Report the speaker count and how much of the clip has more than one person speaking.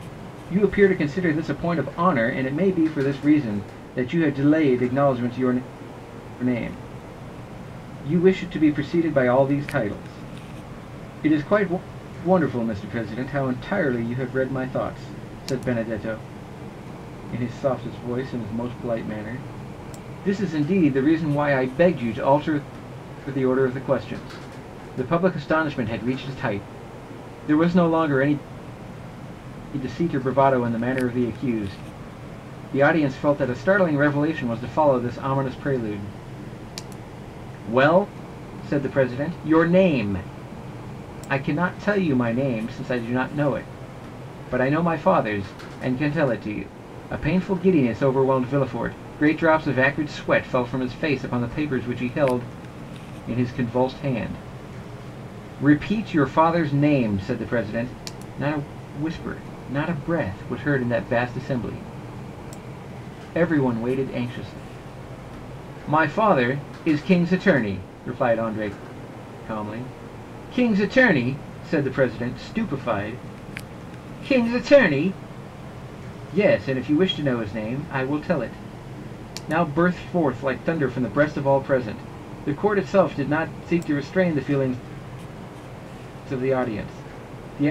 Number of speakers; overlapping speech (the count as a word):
one, no overlap